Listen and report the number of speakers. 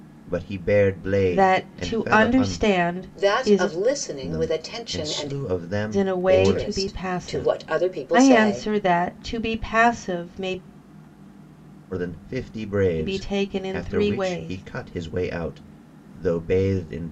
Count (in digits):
3